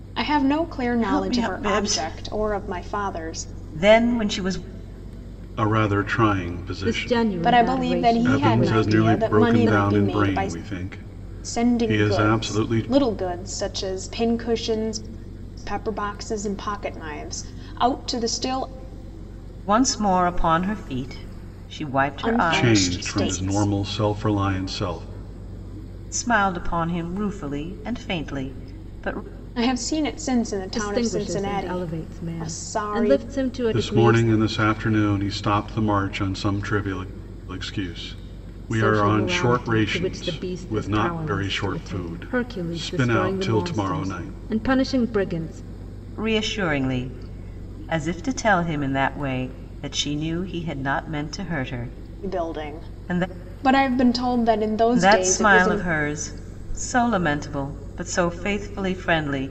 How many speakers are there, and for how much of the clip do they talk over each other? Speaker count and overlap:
four, about 34%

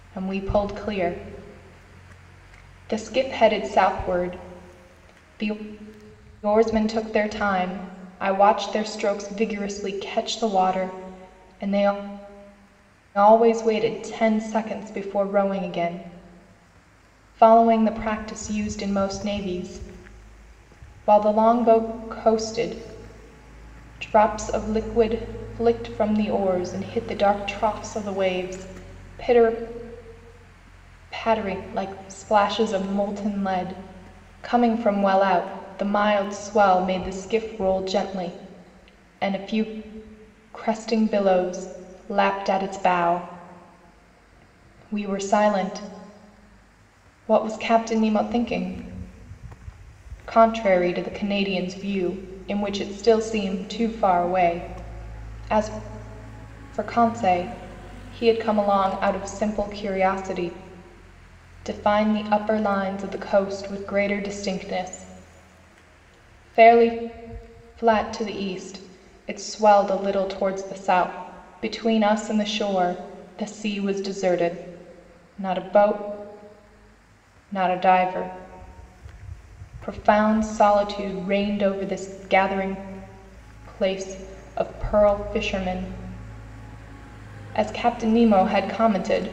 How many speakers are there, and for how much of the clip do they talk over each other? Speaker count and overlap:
one, no overlap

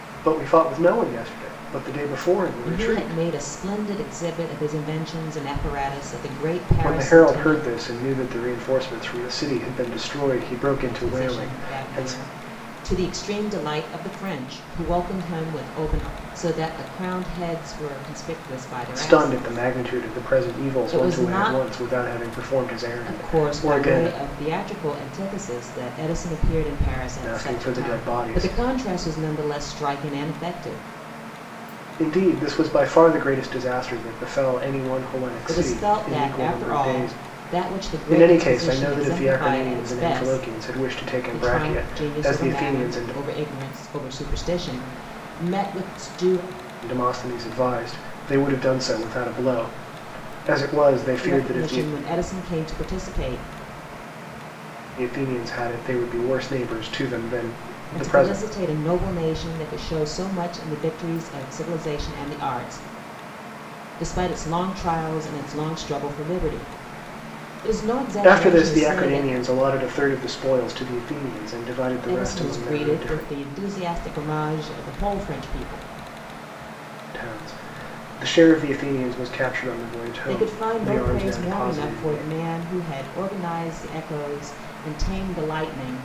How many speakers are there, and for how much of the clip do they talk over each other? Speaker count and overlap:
two, about 23%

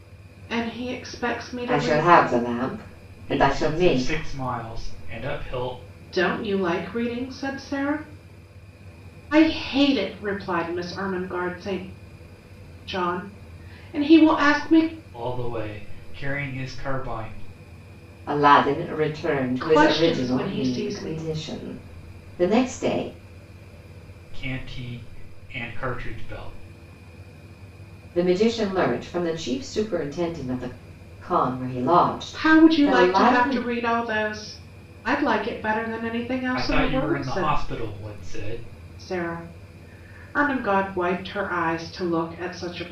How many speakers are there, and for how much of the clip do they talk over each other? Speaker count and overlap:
three, about 13%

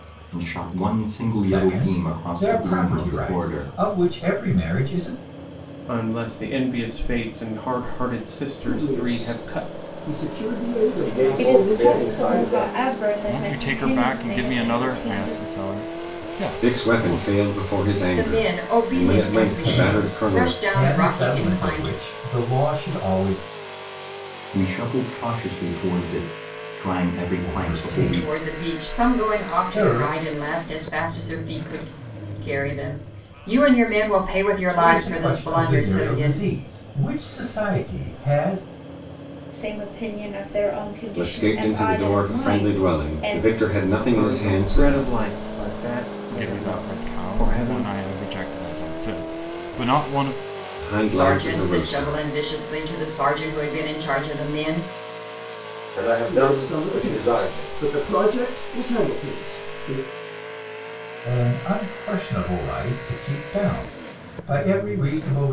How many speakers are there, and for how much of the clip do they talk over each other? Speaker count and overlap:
nine, about 37%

